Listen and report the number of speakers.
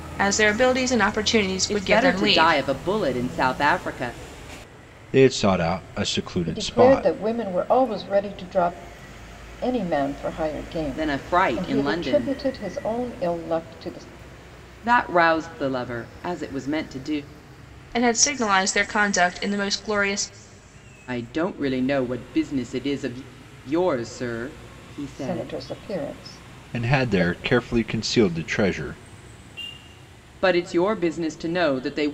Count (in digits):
4